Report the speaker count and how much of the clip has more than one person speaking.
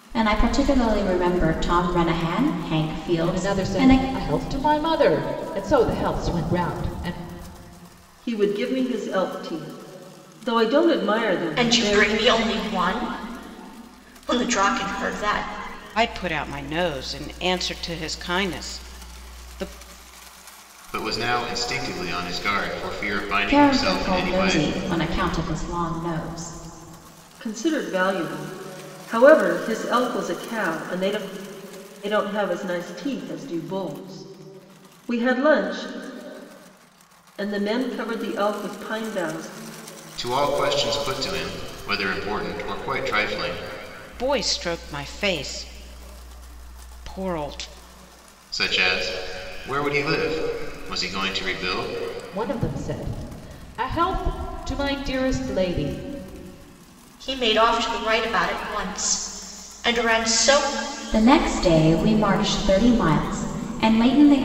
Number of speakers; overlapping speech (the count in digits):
6, about 4%